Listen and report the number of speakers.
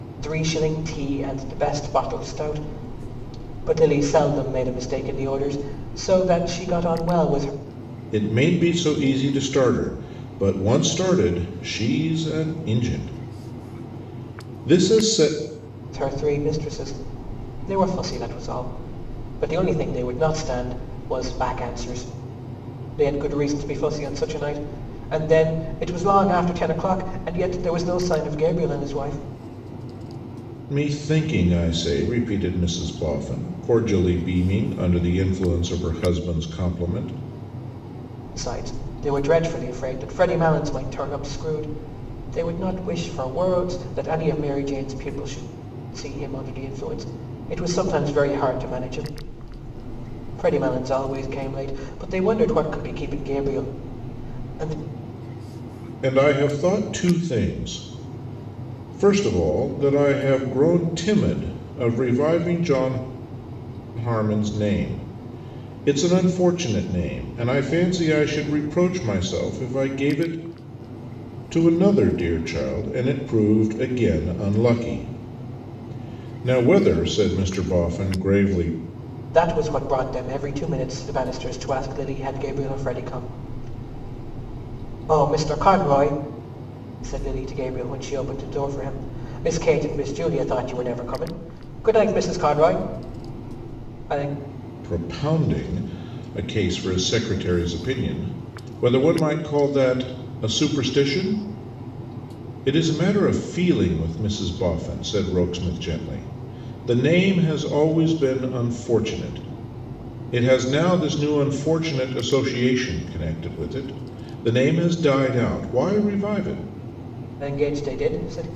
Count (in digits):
2